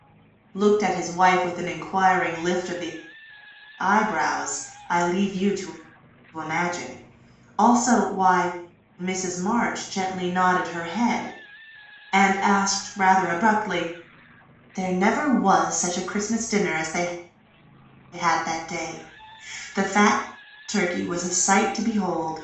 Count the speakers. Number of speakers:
1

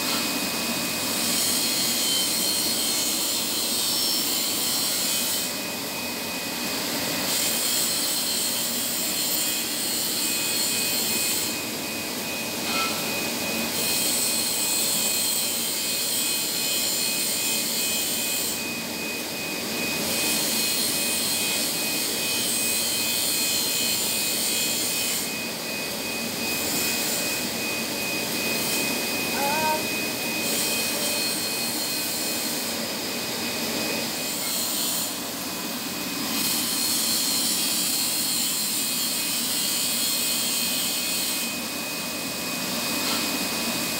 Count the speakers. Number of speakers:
0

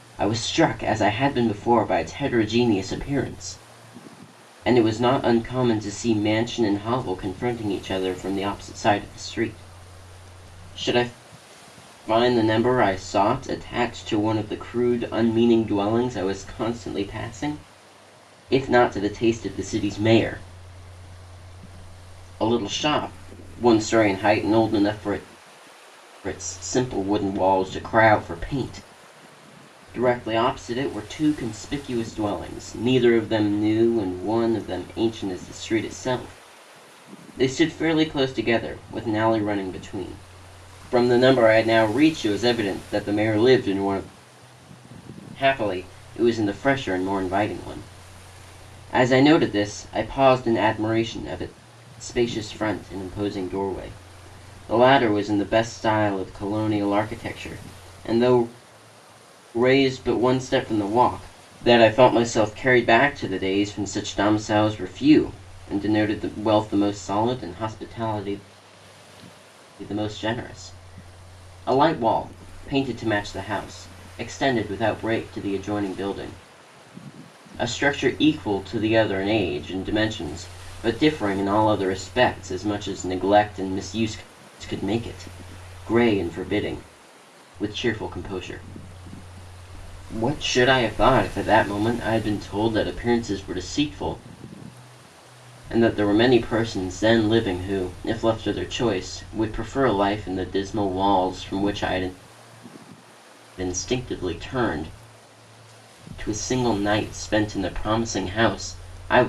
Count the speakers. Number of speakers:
1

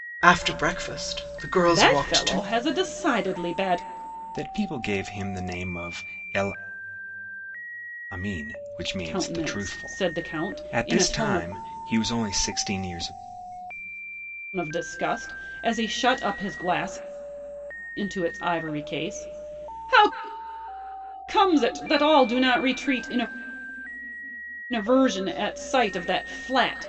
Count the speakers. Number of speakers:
3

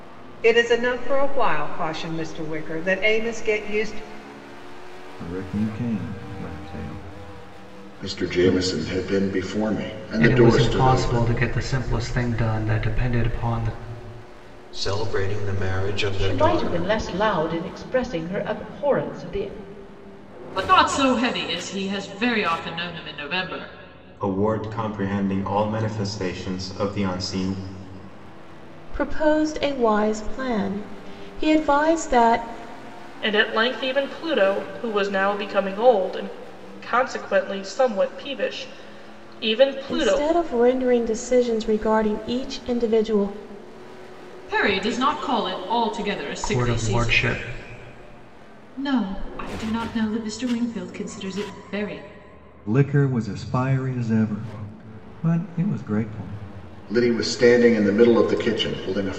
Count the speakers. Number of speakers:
10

